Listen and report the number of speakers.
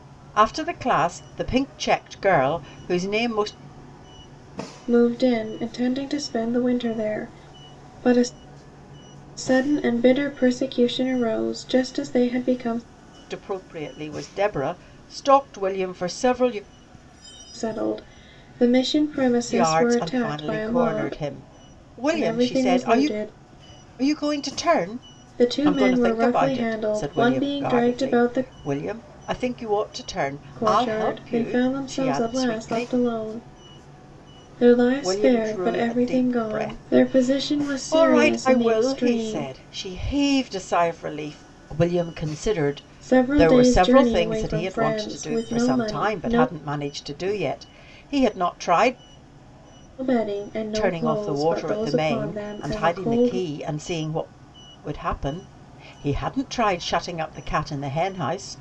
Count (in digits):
2